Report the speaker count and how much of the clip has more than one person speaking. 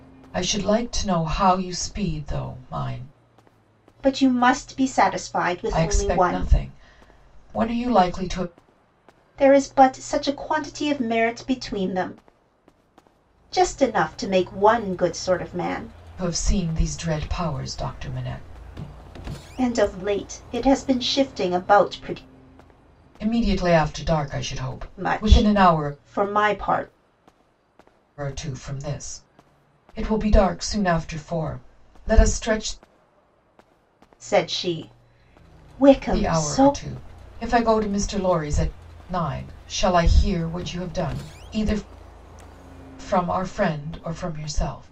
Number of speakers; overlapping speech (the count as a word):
two, about 5%